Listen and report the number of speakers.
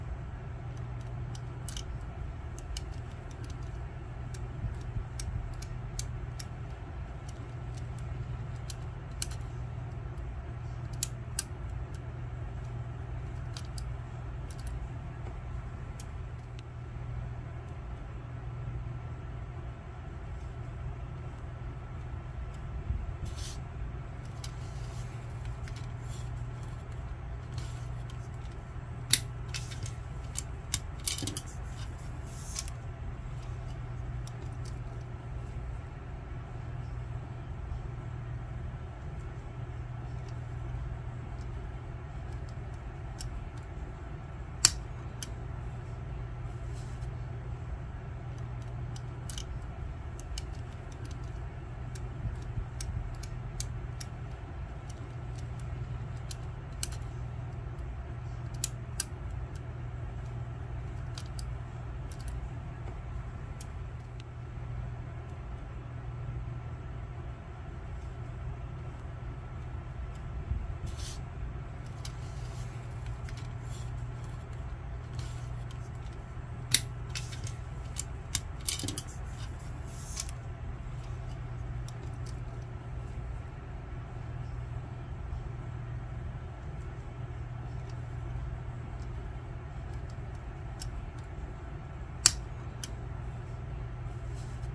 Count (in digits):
0